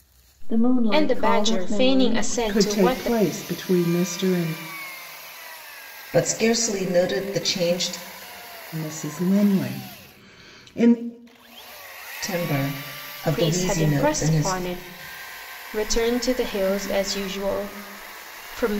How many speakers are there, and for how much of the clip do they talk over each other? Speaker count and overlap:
4, about 19%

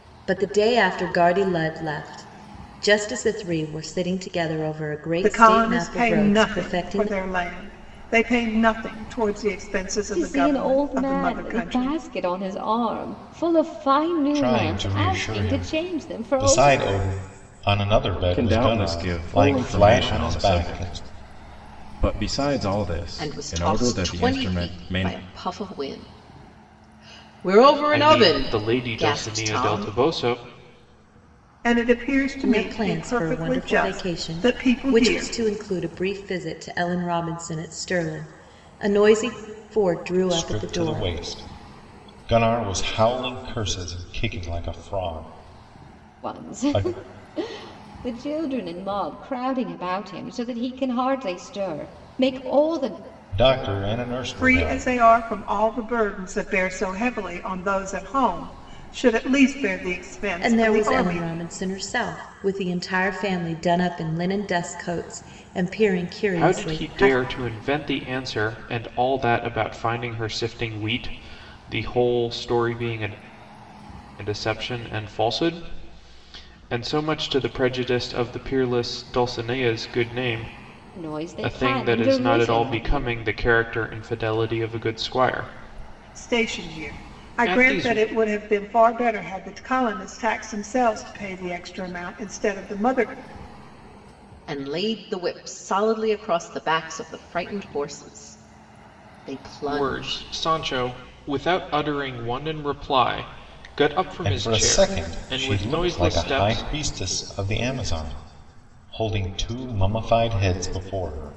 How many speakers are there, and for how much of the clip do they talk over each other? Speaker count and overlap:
7, about 24%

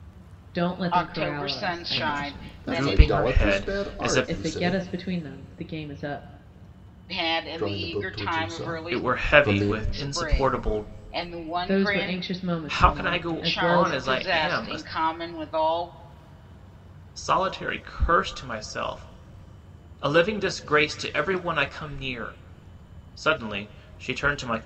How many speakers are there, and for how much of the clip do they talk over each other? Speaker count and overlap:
4, about 40%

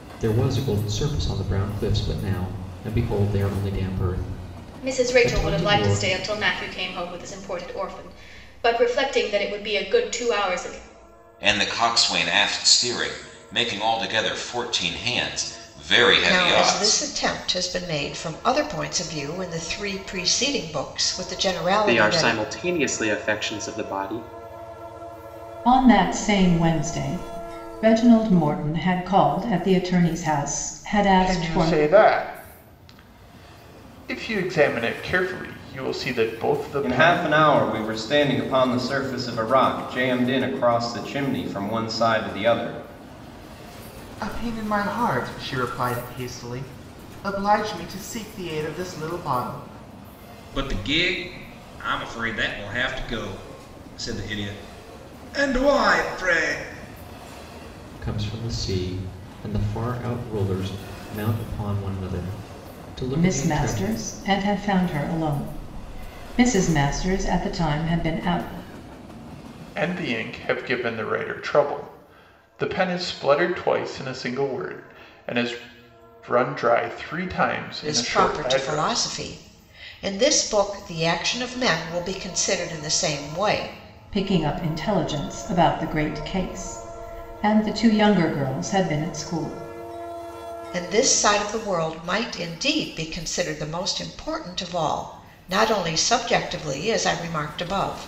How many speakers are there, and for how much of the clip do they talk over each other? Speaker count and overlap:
10, about 6%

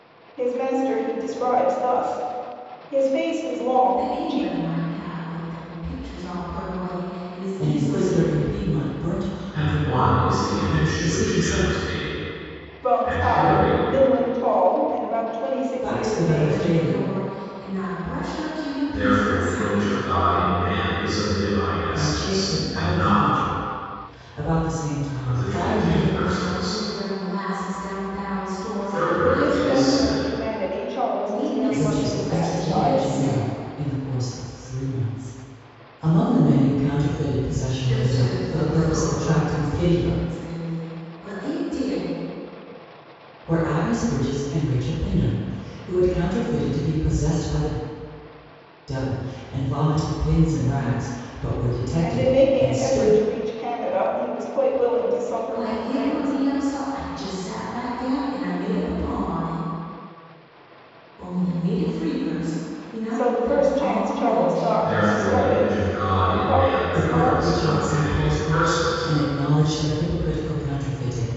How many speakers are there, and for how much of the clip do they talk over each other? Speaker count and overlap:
4, about 35%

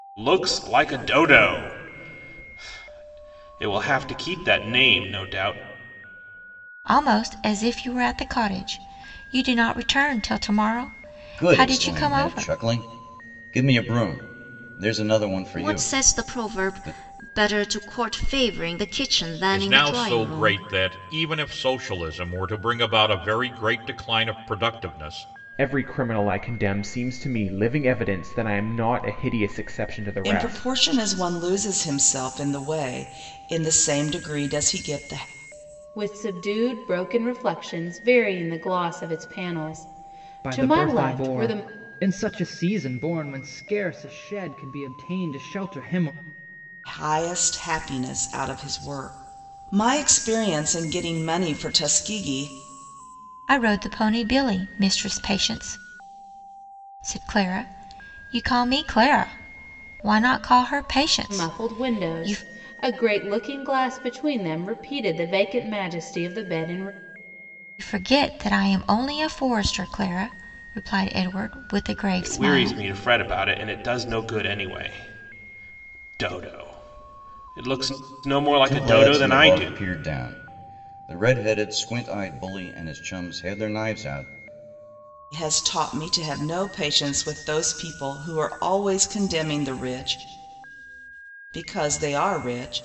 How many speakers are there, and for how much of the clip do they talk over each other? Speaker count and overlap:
9, about 9%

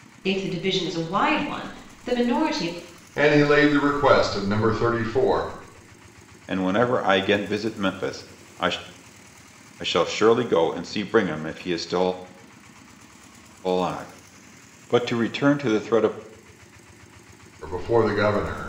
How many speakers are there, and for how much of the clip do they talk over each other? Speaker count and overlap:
3, no overlap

